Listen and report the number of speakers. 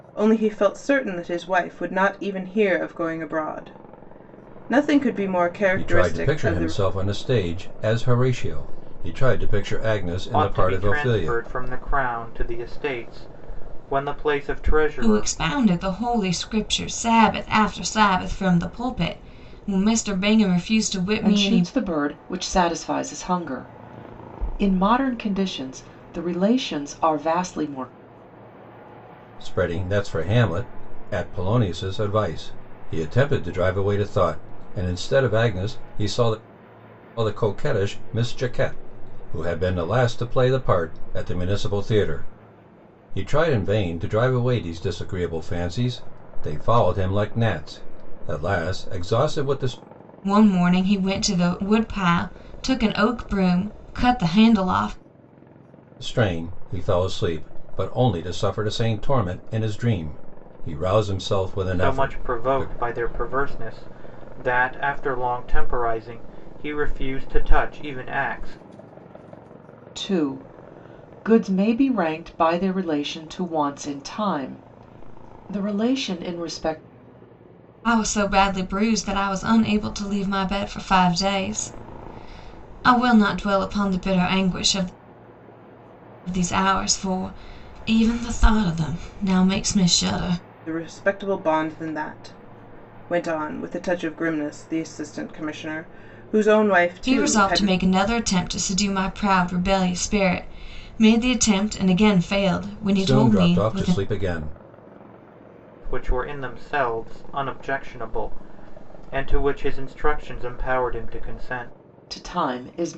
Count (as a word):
five